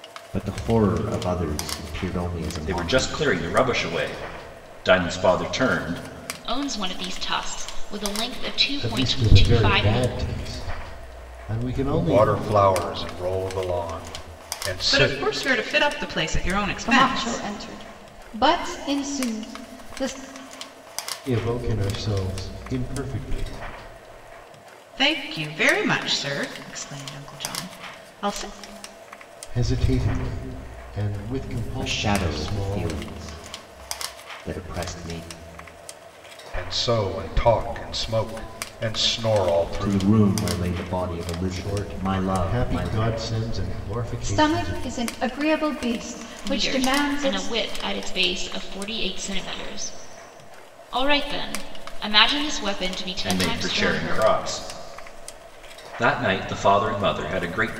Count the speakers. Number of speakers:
7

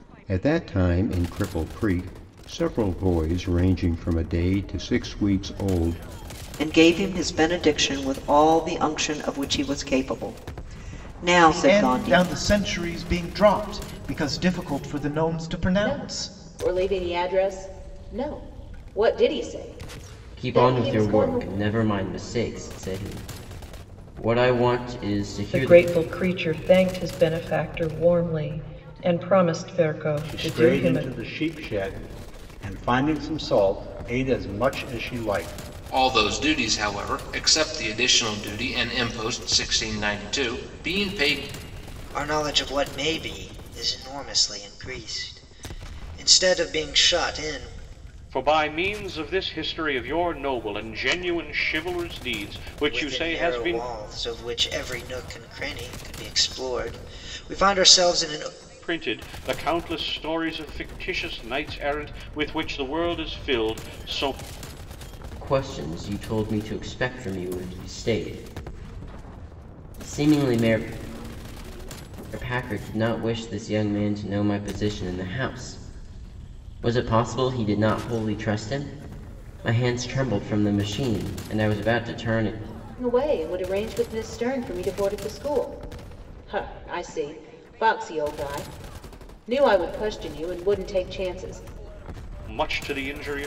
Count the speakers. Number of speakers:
10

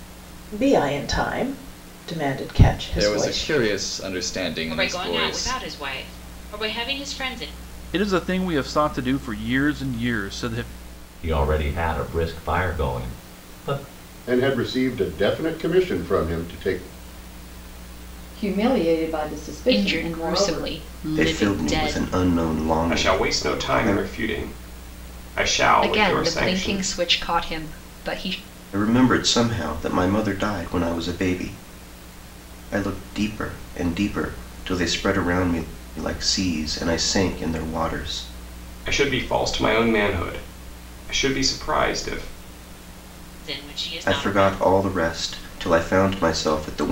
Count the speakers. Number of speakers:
10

